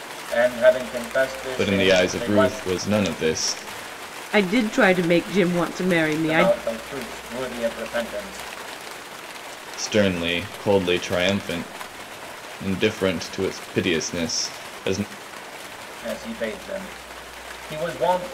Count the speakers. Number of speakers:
3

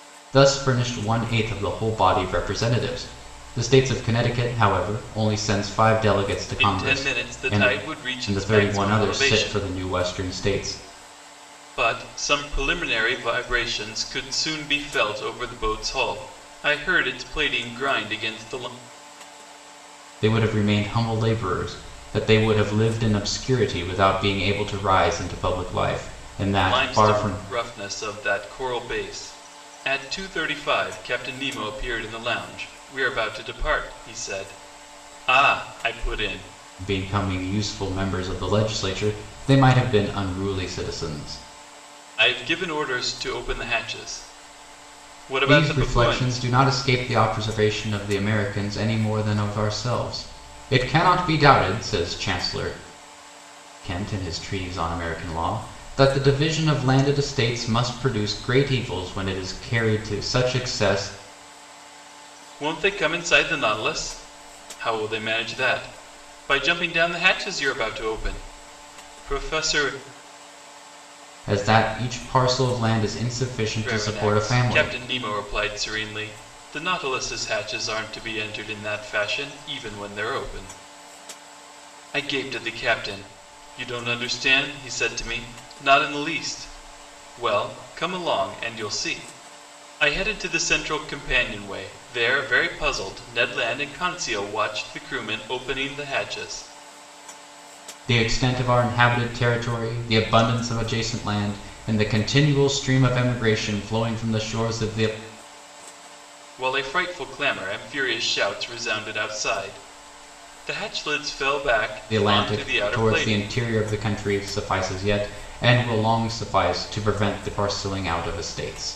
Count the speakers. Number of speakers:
2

